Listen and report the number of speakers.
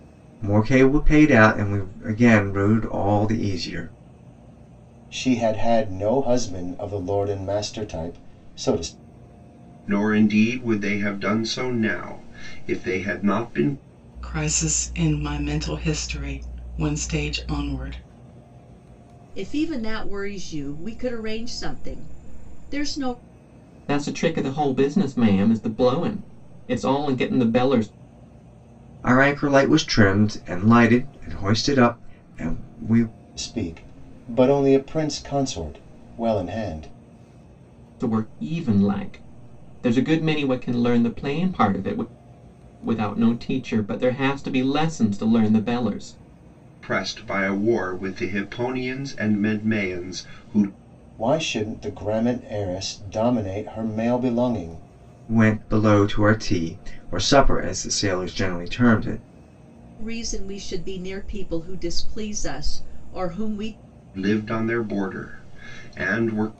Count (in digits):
6